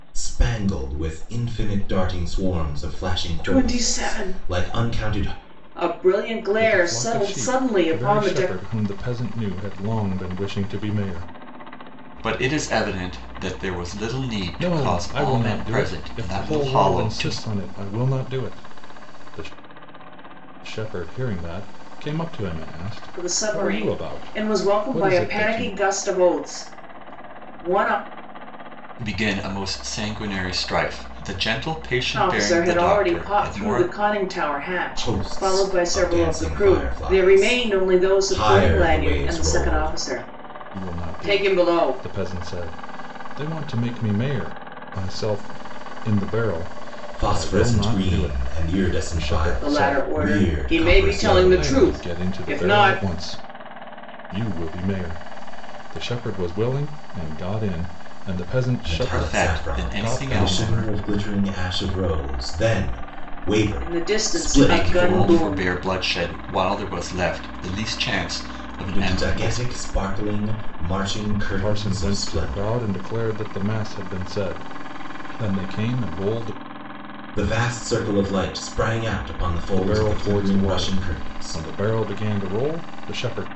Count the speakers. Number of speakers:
four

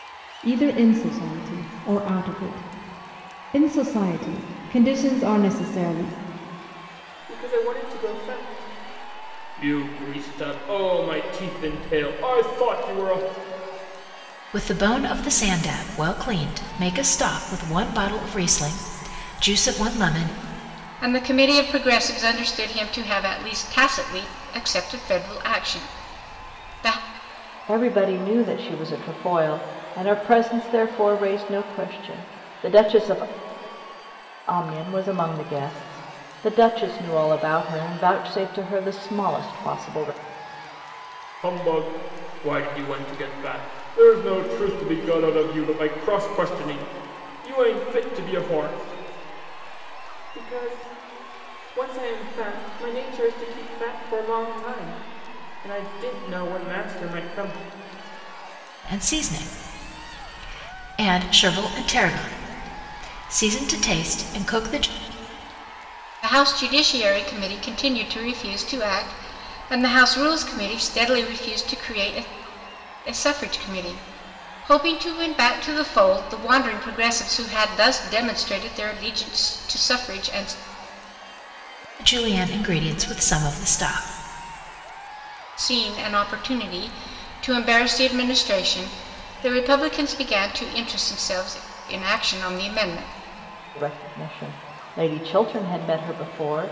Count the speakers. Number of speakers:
five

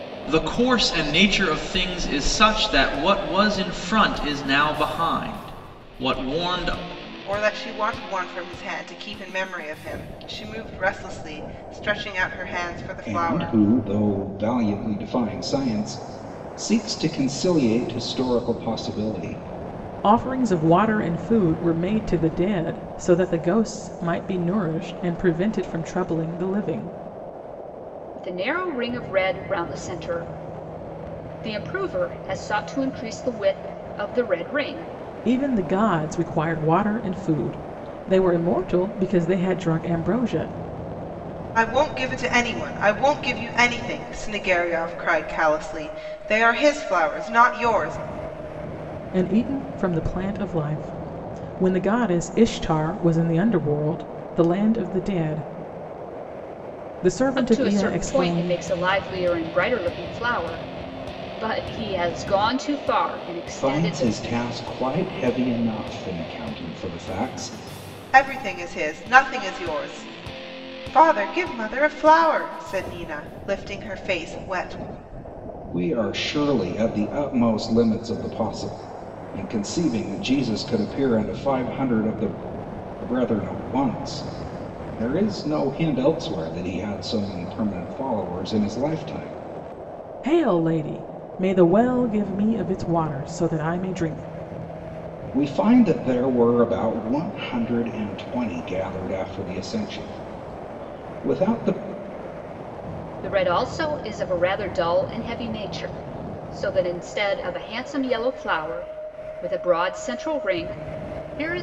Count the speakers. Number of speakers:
five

